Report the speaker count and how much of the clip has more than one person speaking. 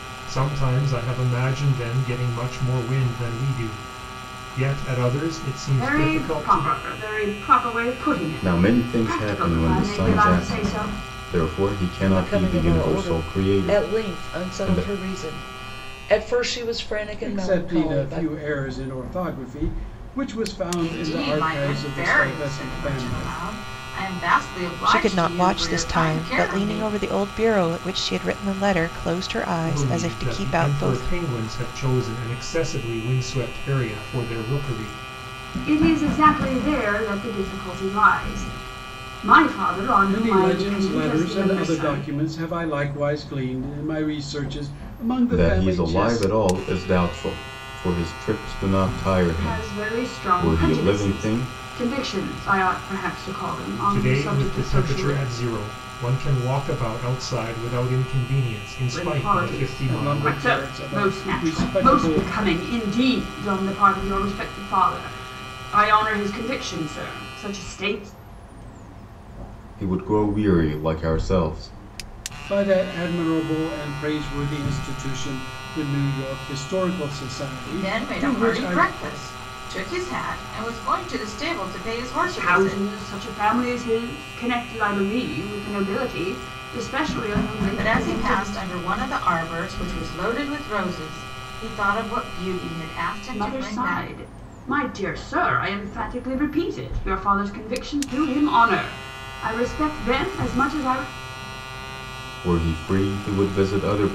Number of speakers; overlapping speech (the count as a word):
seven, about 26%